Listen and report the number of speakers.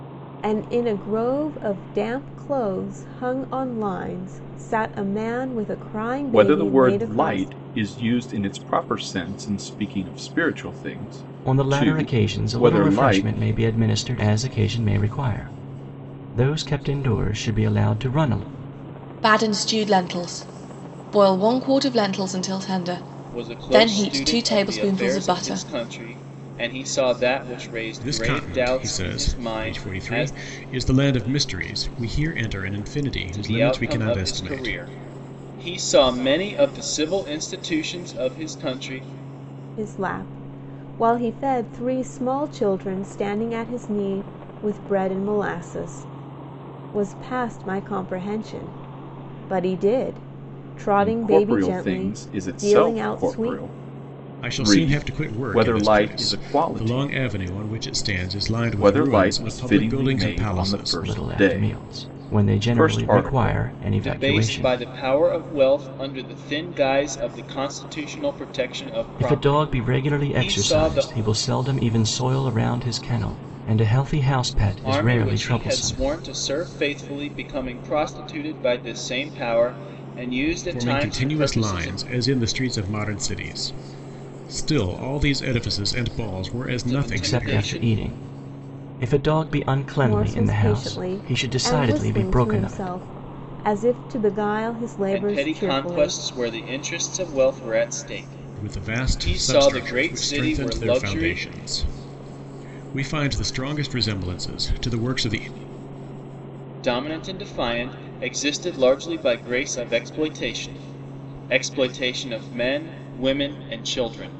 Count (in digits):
6